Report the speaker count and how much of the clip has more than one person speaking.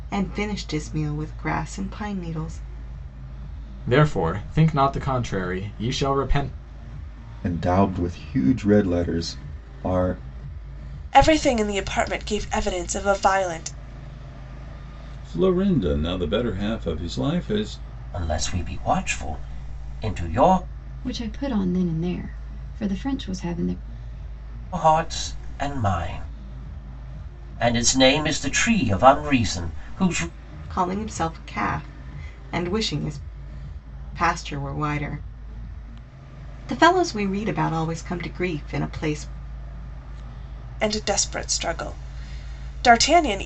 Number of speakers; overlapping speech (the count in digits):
7, no overlap